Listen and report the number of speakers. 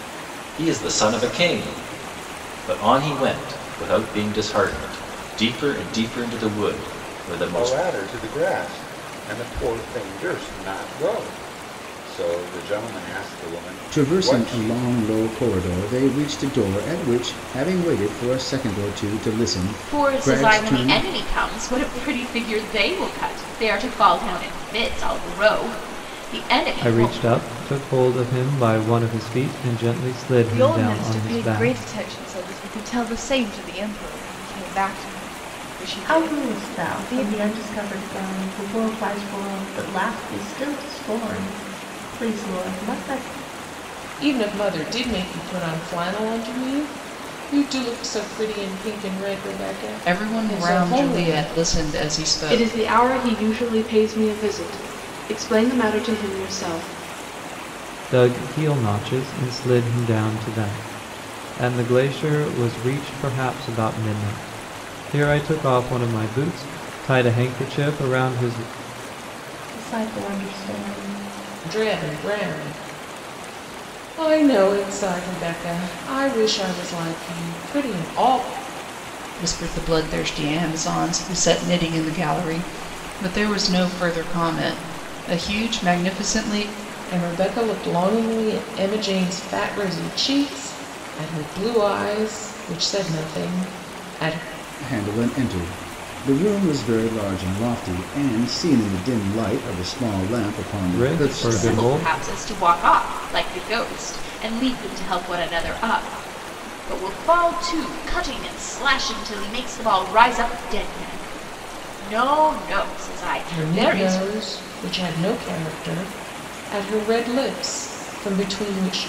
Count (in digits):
10